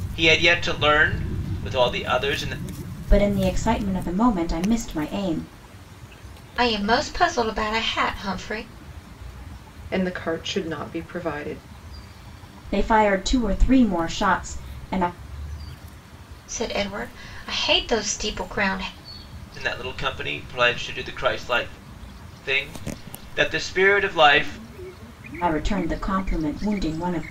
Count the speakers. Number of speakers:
four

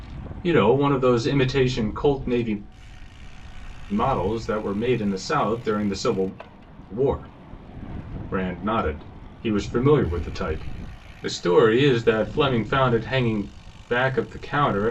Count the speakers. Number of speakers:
one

